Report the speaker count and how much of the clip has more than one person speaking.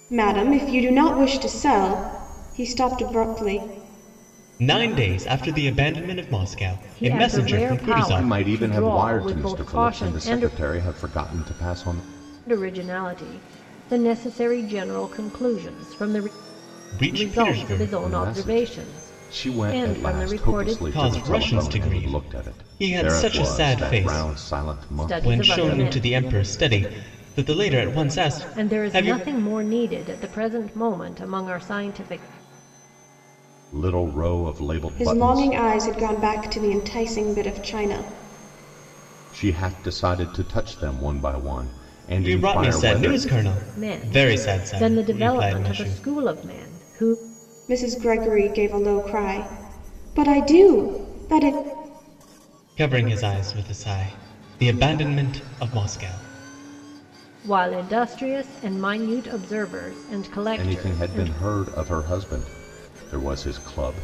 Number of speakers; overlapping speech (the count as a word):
four, about 27%